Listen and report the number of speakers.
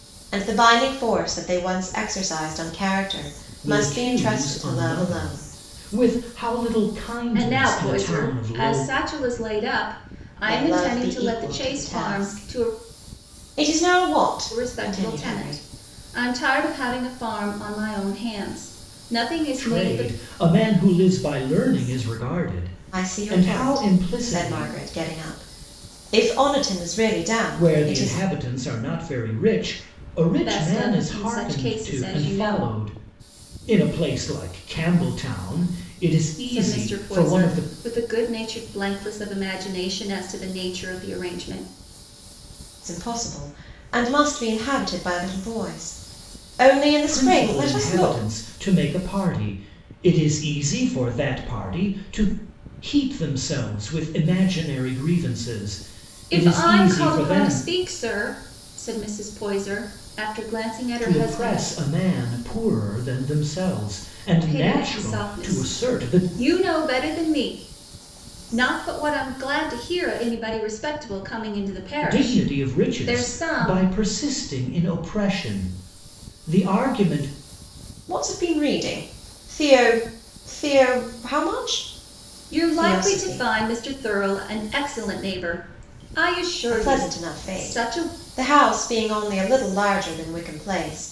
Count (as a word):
three